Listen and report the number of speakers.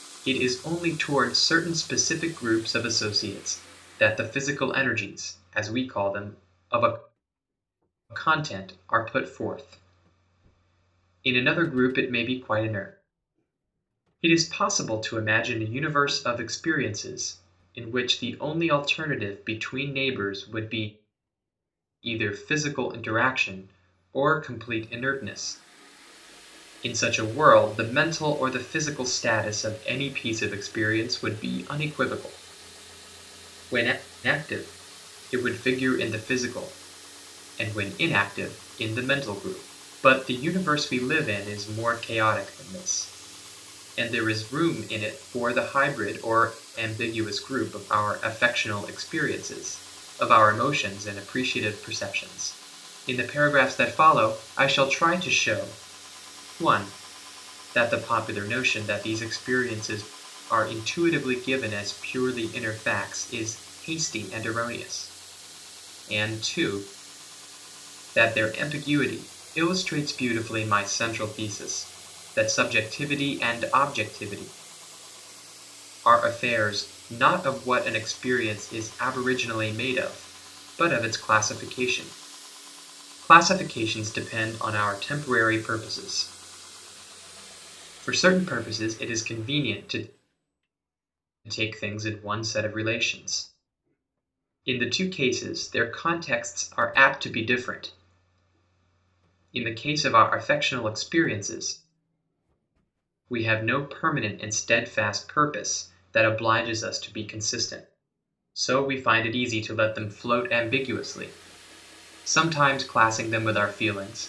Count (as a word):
one